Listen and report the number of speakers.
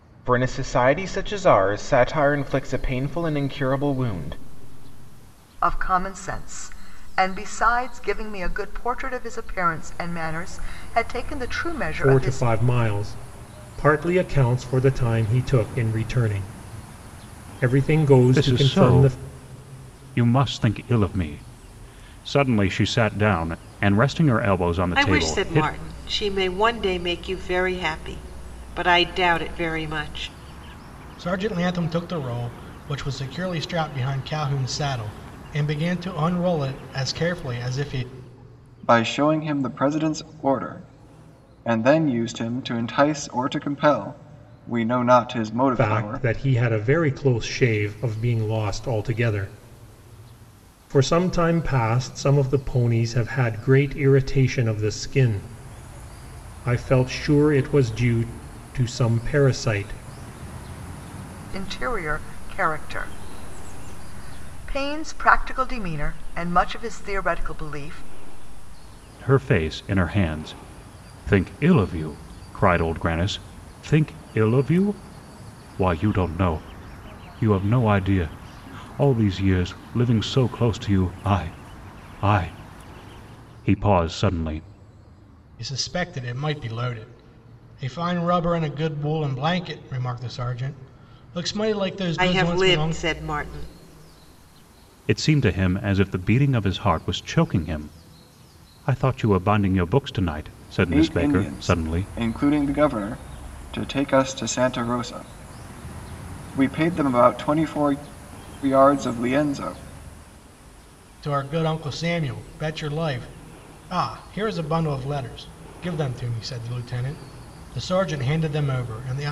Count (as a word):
seven